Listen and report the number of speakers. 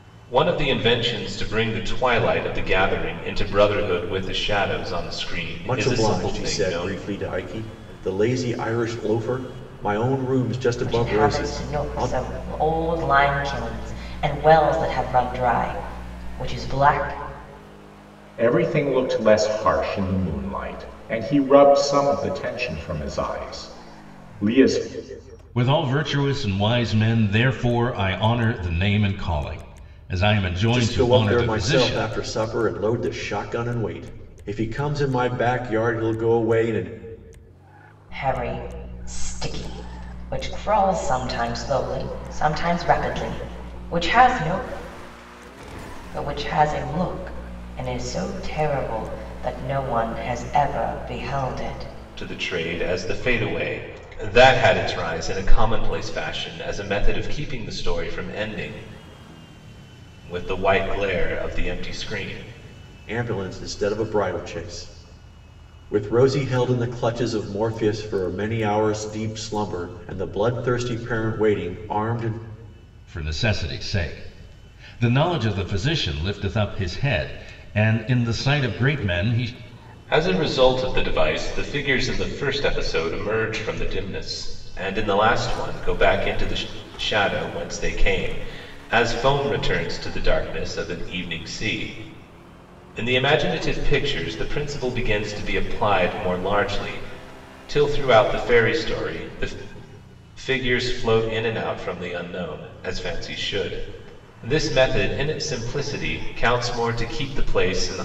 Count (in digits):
5